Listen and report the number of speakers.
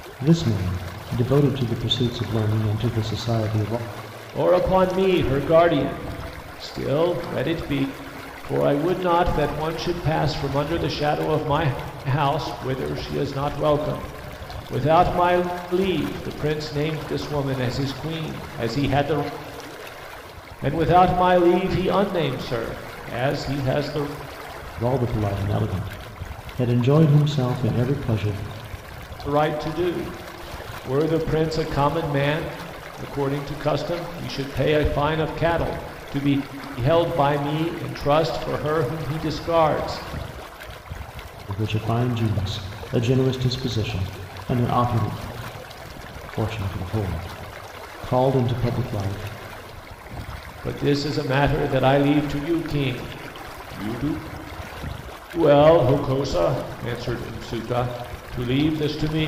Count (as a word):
two